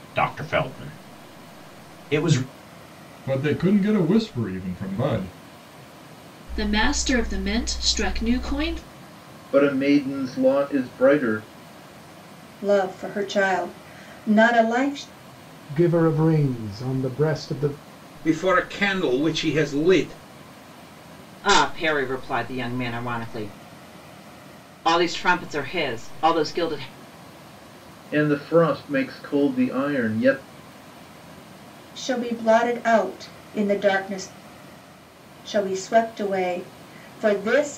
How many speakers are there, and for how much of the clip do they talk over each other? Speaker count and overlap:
eight, no overlap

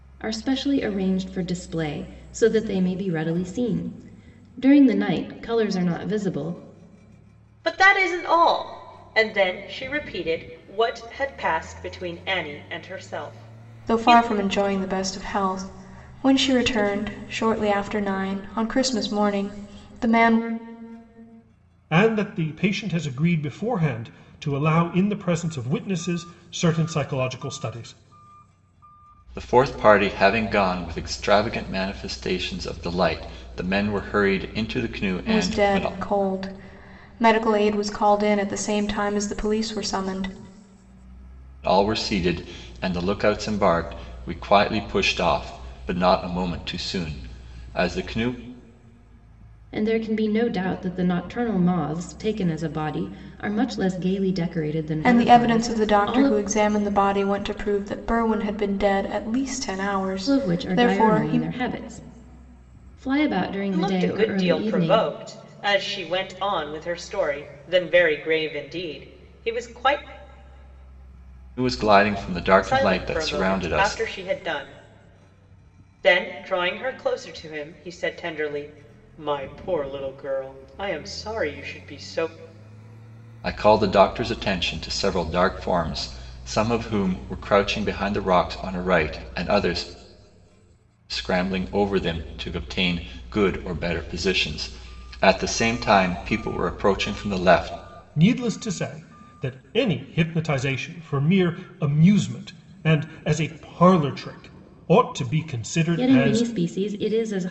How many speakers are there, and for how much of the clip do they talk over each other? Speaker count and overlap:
five, about 6%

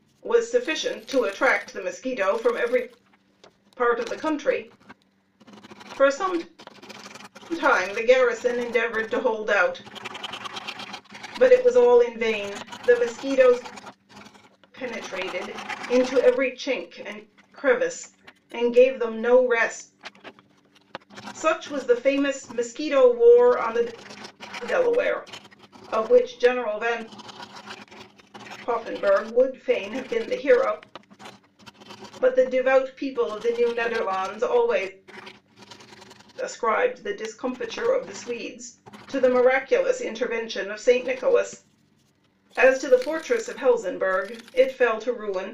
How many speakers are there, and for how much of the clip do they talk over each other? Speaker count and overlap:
one, no overlap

